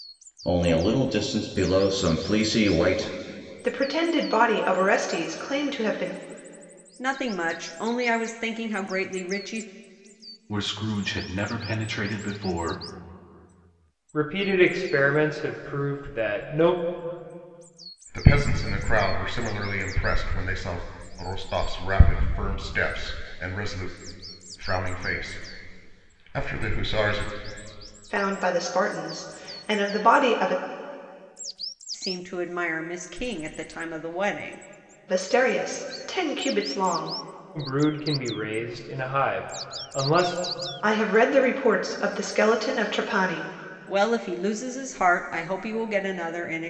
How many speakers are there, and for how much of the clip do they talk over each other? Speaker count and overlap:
six, no overlap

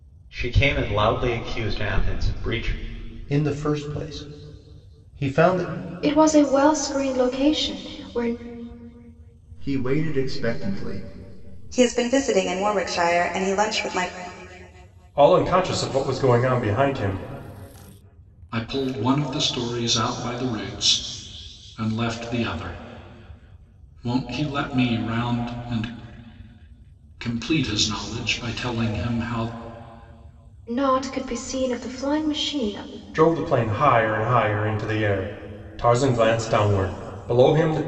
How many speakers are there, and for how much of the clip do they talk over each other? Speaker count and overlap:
seven, no overlap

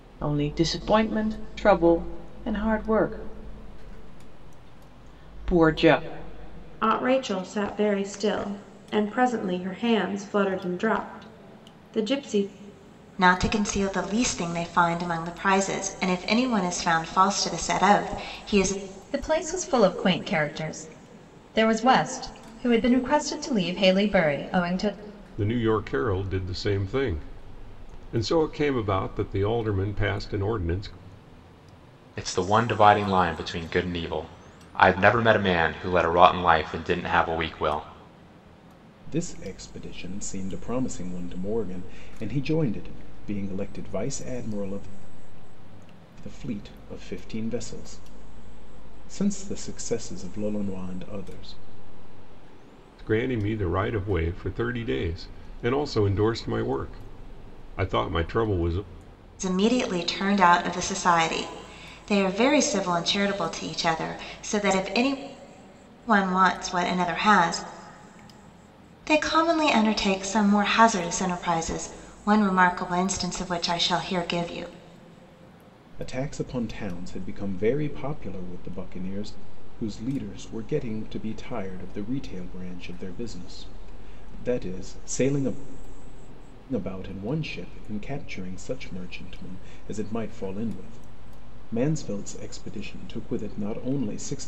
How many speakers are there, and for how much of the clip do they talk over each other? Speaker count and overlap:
seven, no overlap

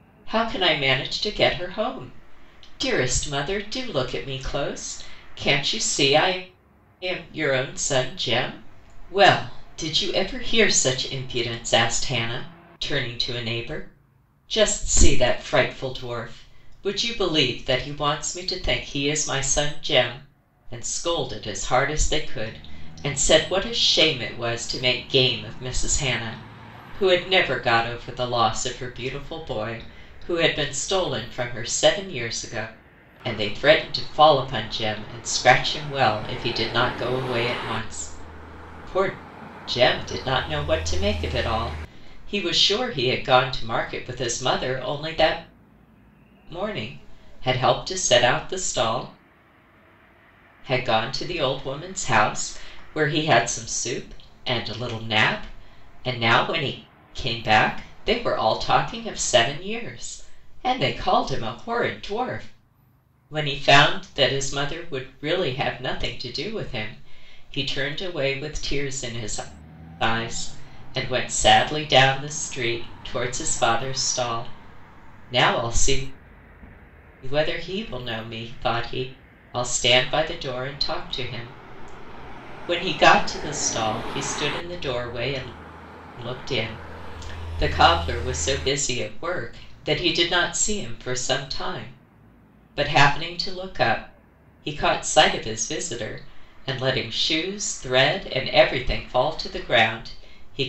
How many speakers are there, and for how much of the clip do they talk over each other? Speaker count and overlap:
one, no overlap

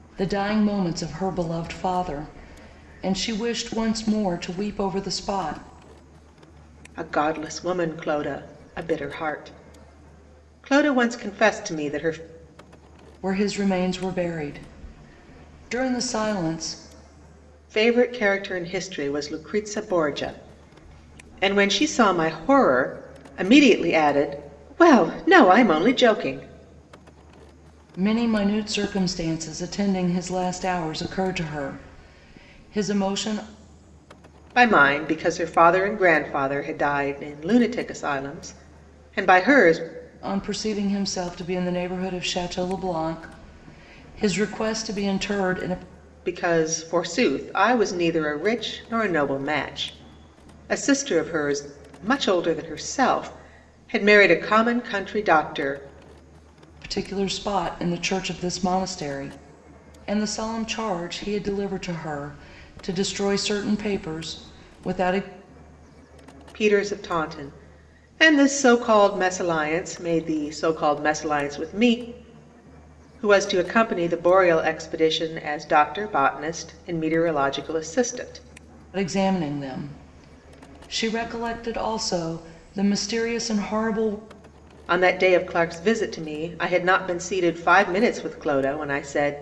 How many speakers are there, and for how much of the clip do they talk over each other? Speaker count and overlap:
two, no overlap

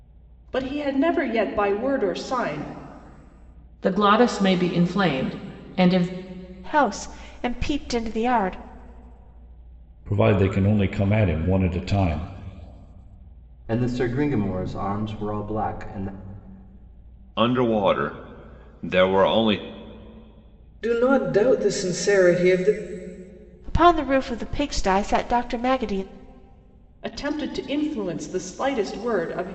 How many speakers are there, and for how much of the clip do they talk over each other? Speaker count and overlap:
seven, no overlap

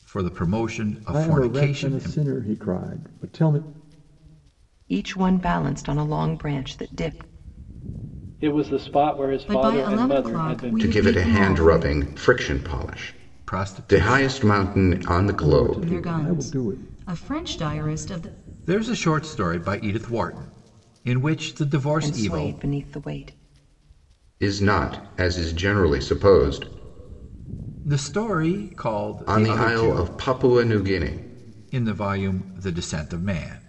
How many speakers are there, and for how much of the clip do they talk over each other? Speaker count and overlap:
six, about 21%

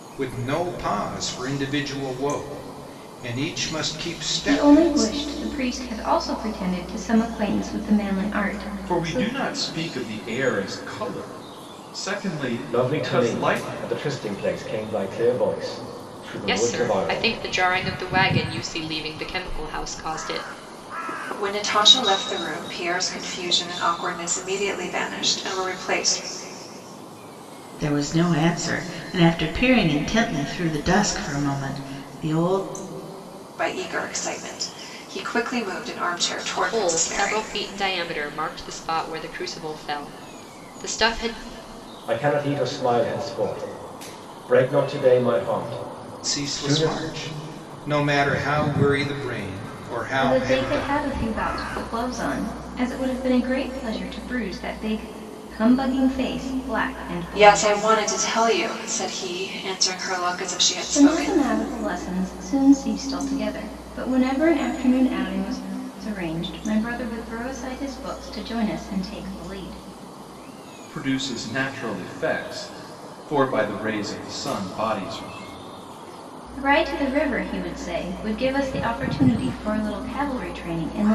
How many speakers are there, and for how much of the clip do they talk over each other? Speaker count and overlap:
seven, about 8%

